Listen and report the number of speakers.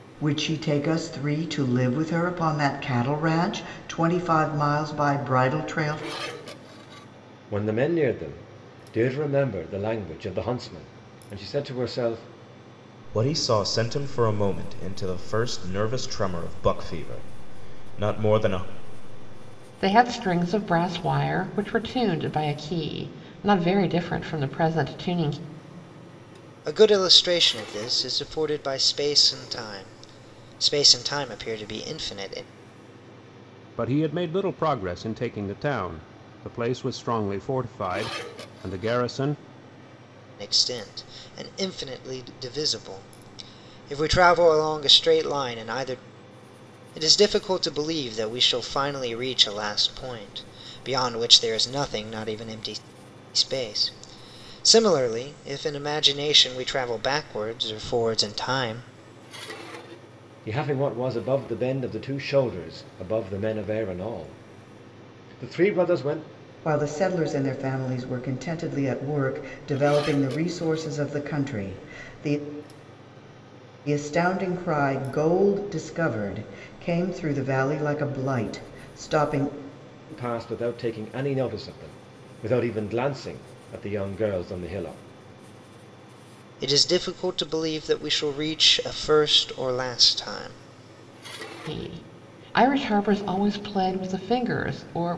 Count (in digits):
6